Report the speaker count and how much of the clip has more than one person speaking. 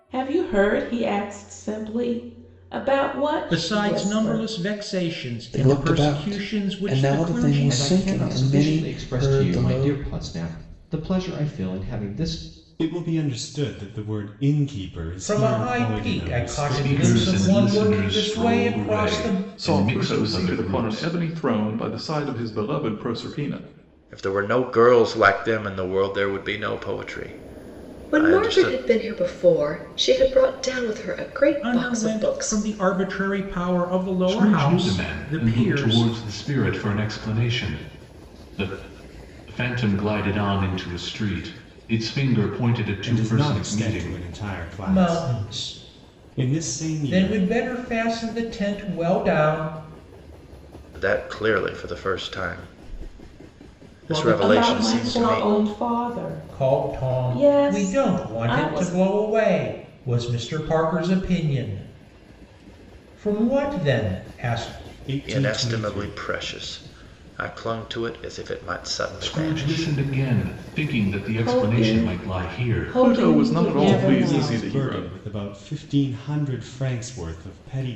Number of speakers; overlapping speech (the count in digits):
10, about 36%